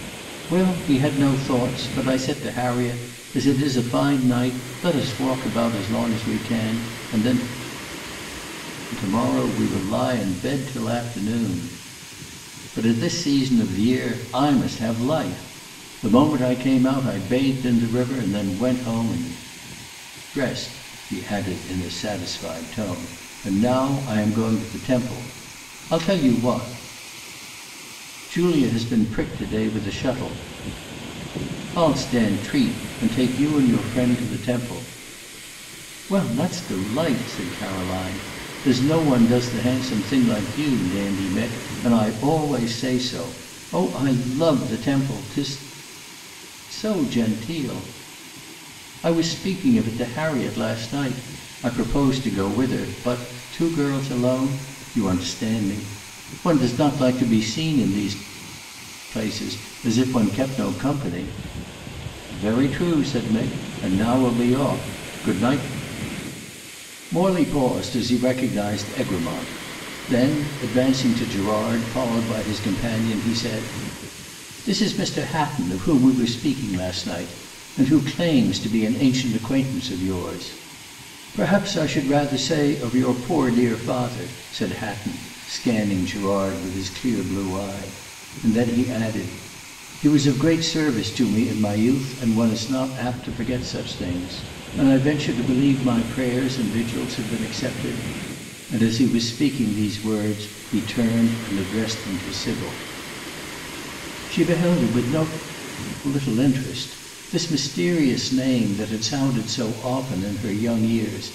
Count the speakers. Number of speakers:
1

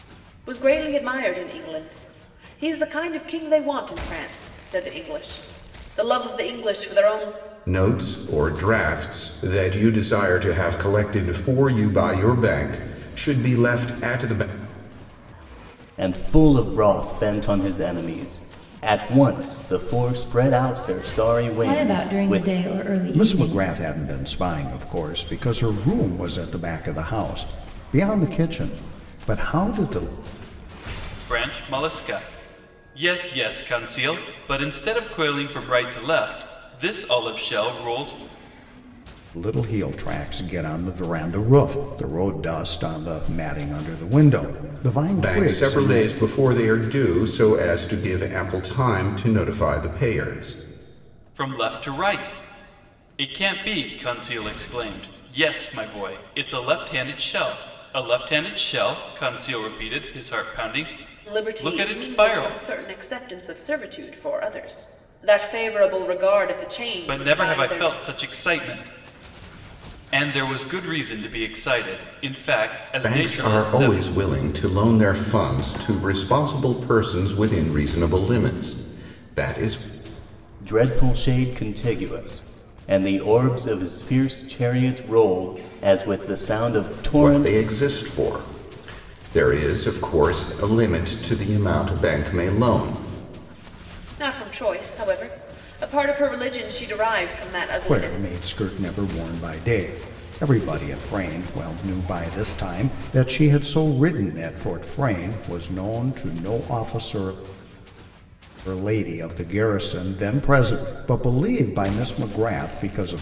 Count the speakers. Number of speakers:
6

